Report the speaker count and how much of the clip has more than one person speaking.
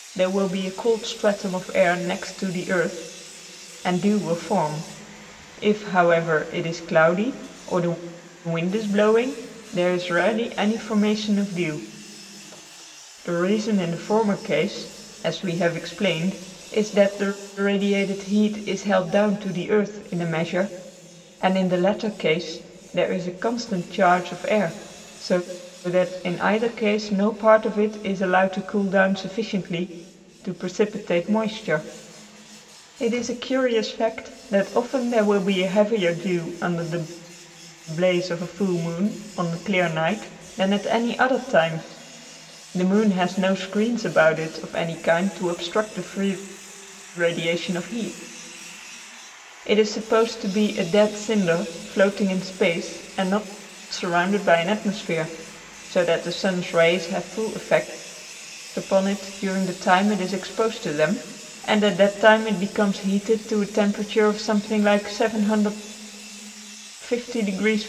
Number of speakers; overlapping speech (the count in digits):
1, no overlap